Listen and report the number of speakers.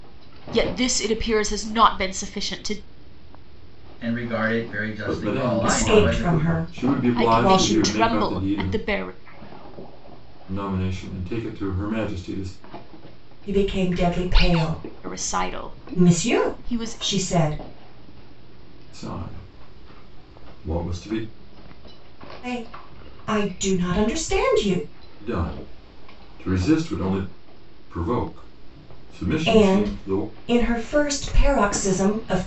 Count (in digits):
4